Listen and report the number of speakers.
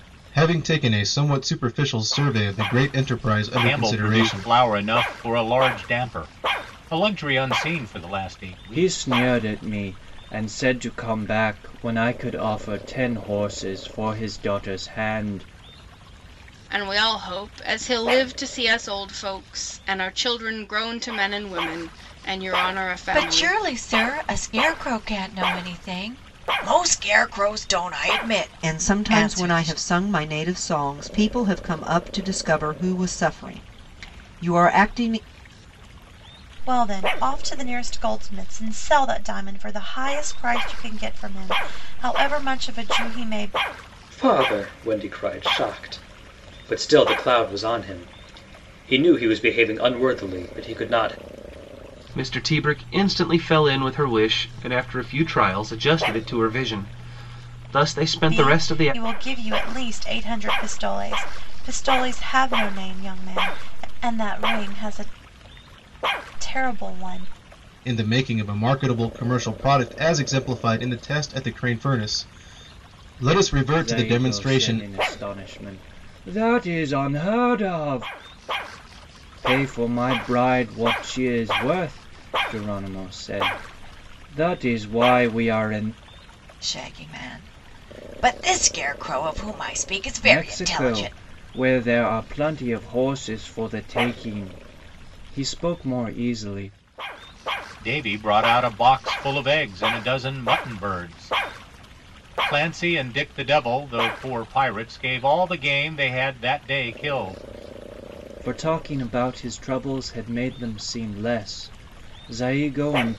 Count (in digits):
9